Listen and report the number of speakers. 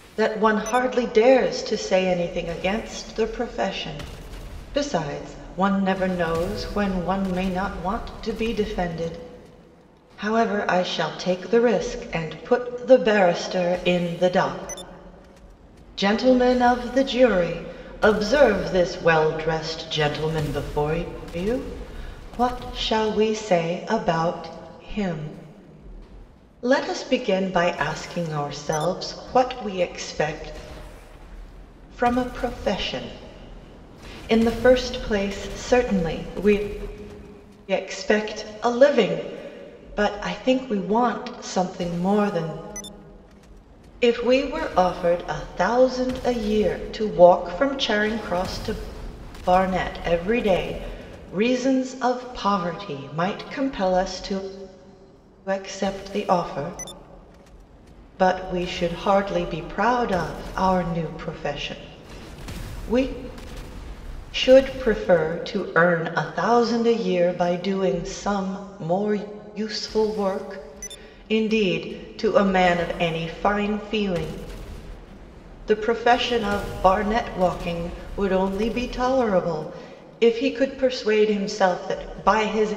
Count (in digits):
1